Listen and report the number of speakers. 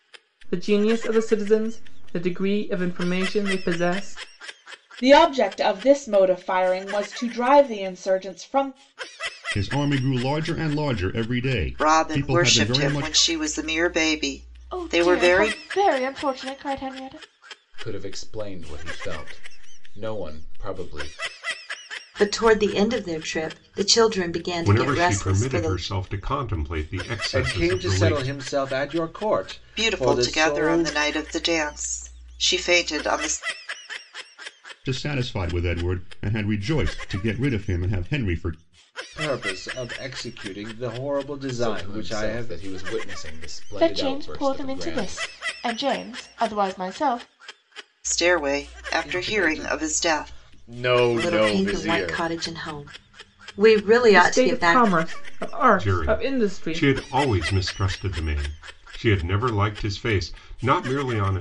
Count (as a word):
nine